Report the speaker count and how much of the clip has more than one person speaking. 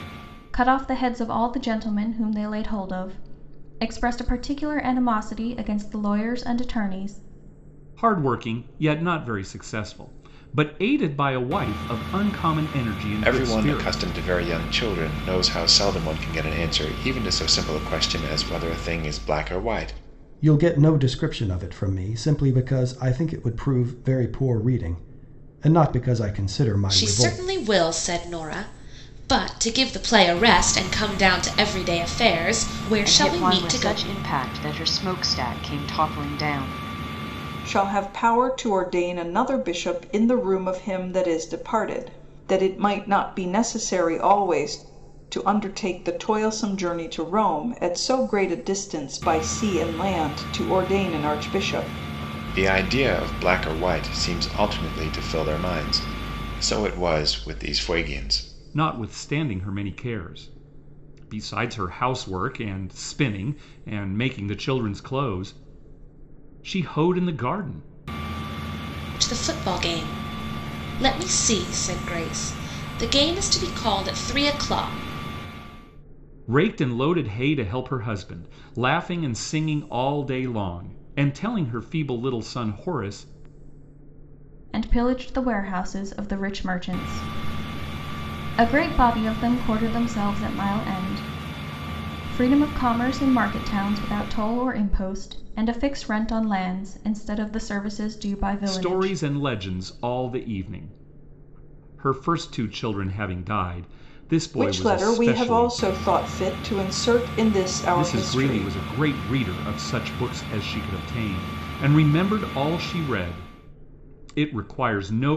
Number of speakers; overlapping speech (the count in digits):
7, about 4%